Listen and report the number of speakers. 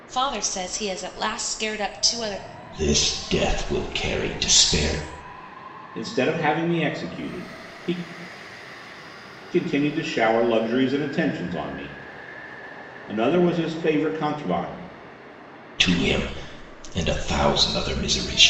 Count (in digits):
3